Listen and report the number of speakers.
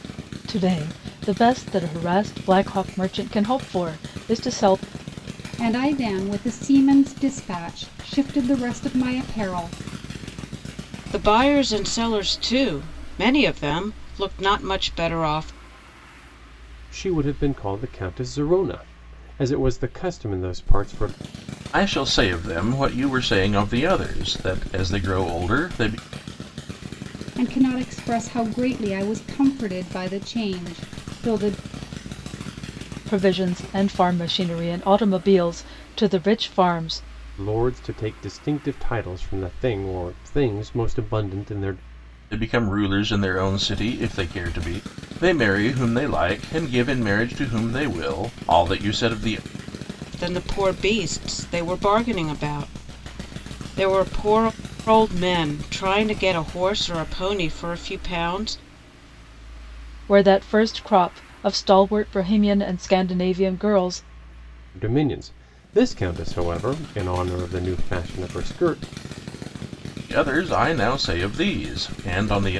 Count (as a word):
five